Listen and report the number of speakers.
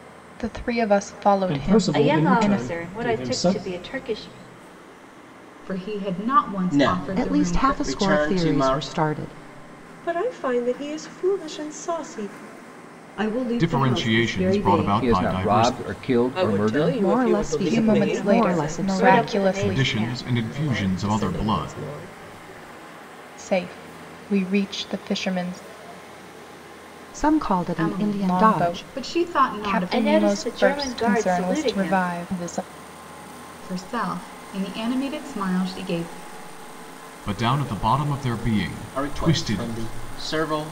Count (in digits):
10